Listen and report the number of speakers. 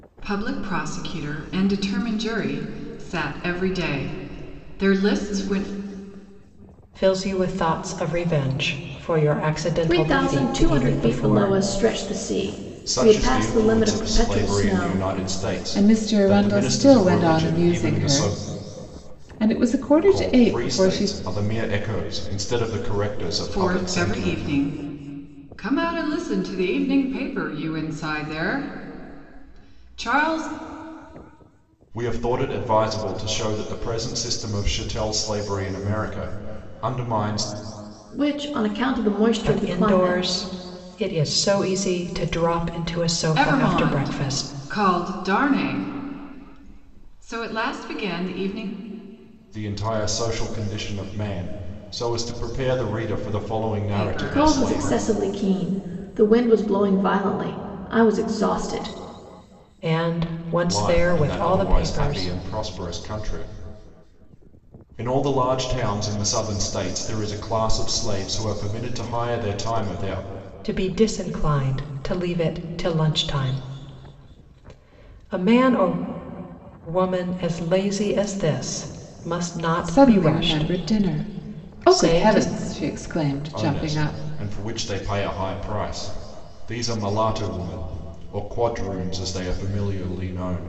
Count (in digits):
5